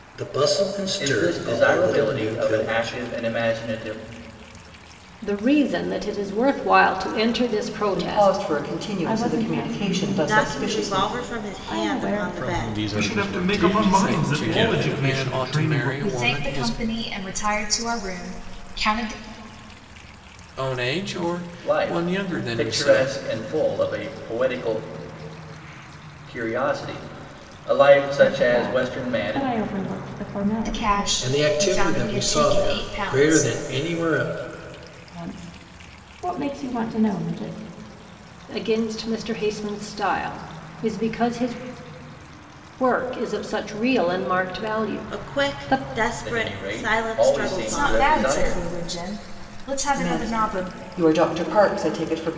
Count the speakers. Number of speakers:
10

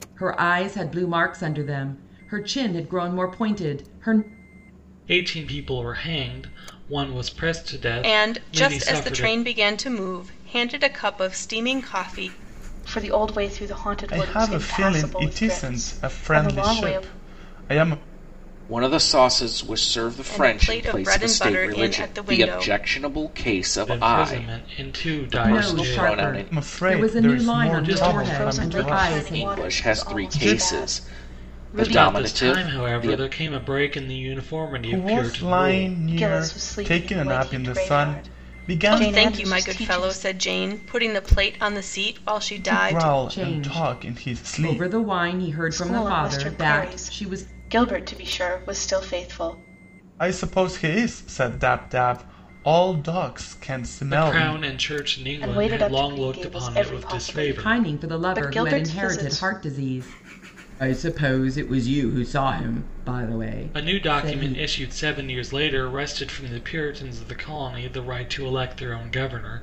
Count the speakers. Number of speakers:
6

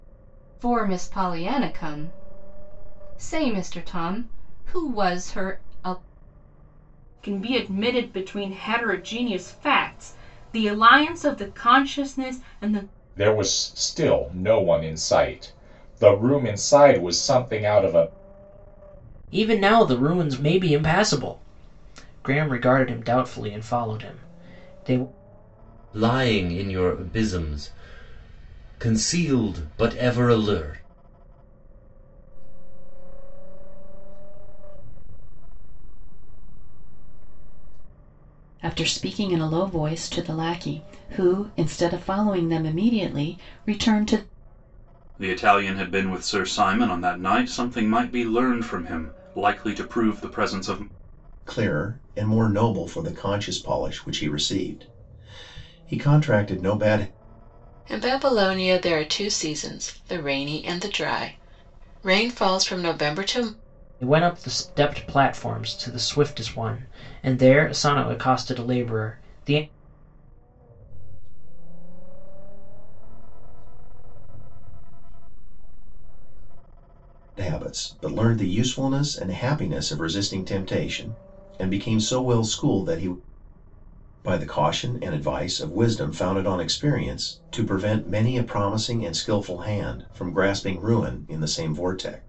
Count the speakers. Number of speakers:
10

